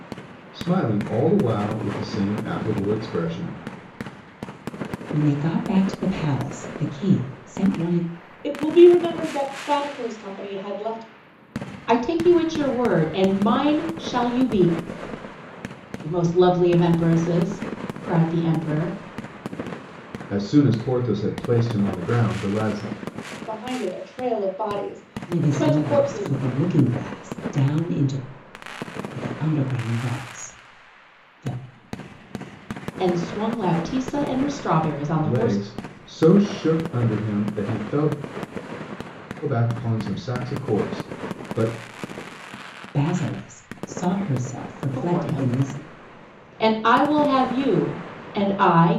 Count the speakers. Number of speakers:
four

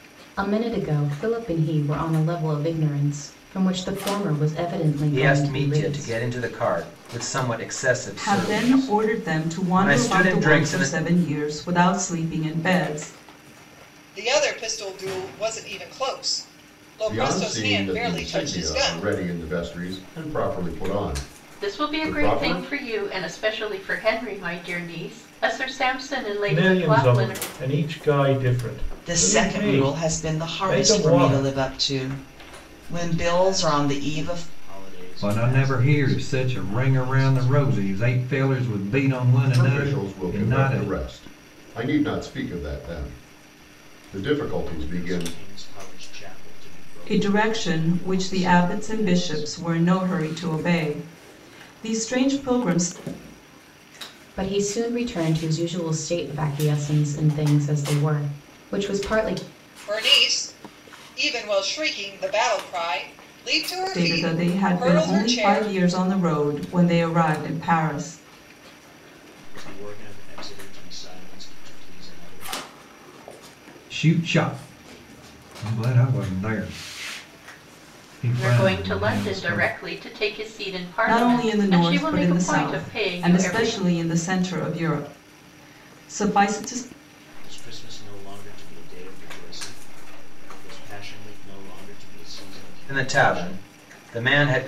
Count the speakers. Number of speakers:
ten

